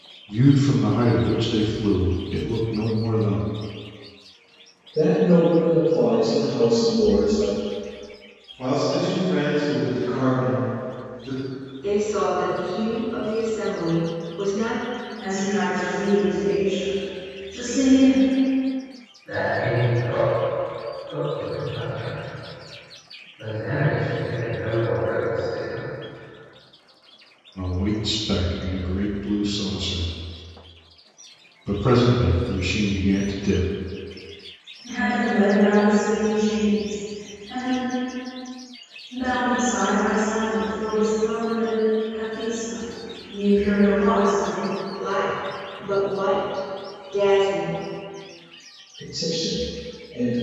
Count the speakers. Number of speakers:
six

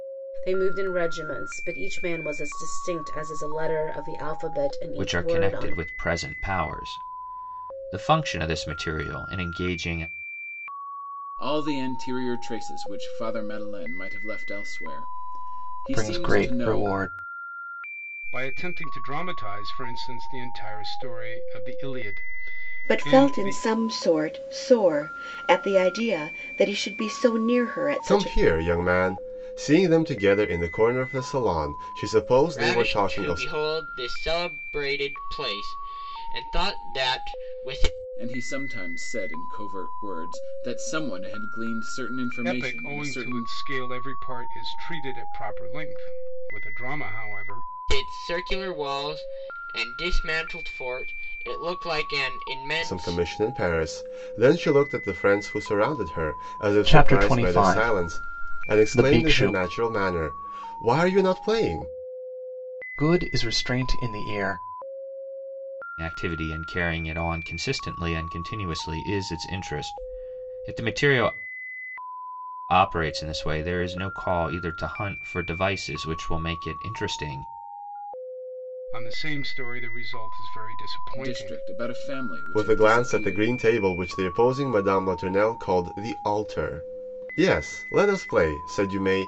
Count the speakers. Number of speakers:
eight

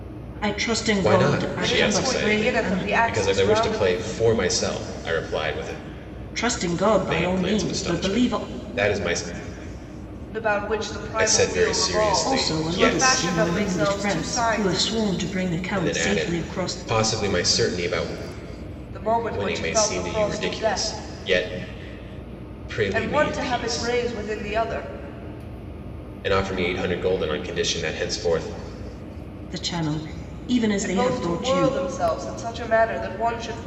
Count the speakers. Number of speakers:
three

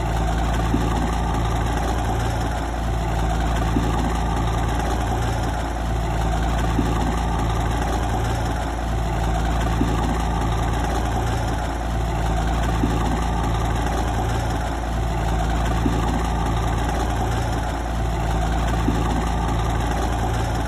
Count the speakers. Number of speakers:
zero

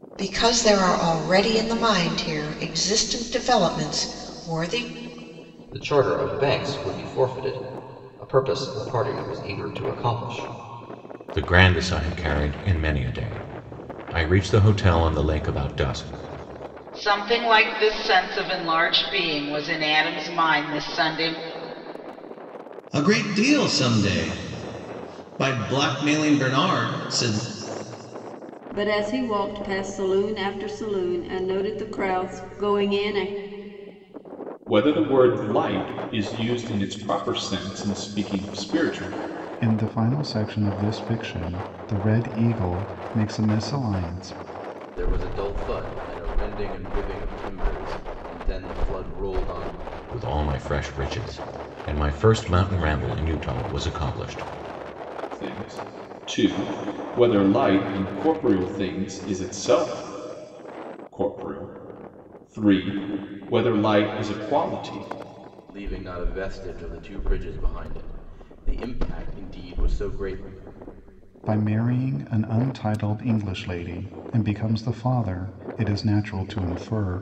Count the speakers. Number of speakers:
nine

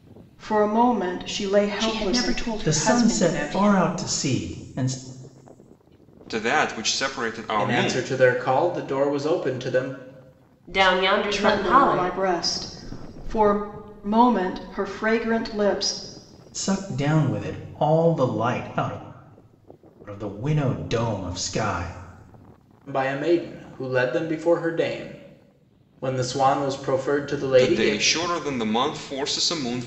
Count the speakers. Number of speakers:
six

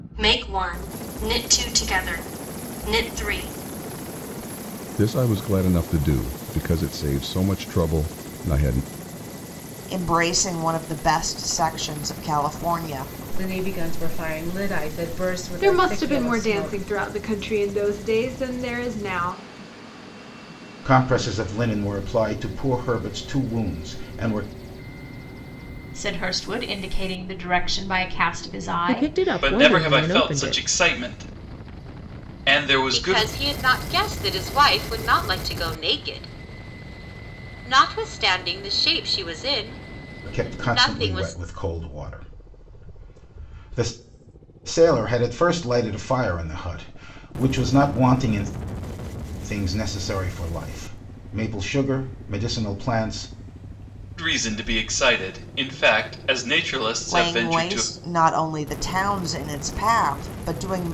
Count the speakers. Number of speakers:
ten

